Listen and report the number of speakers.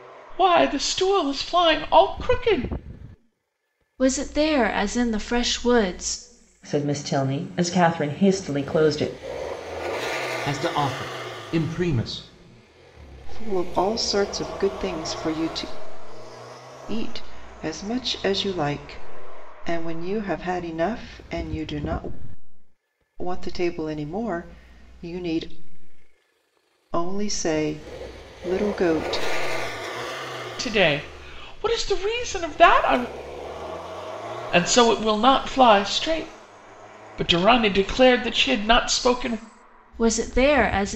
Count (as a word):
five